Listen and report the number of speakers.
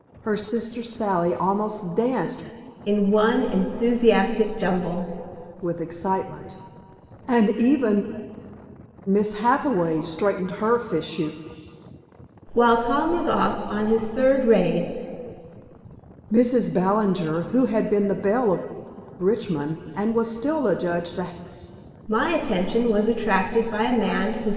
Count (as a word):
two